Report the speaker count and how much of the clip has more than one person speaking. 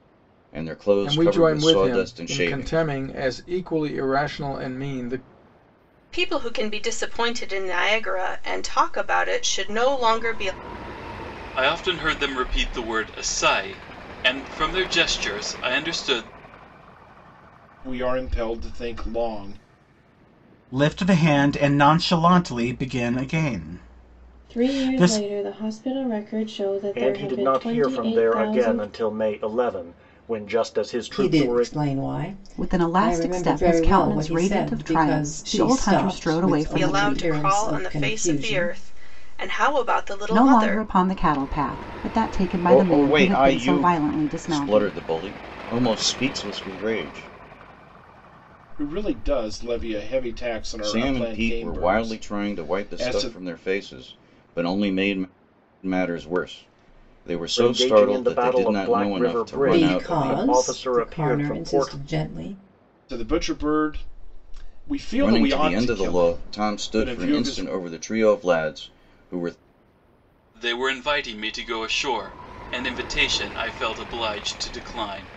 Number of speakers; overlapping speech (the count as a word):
ten, about 32%